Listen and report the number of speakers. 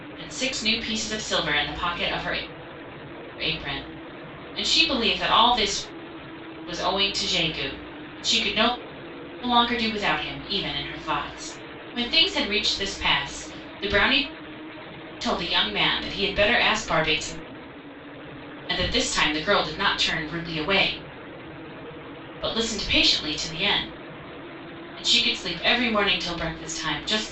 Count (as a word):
one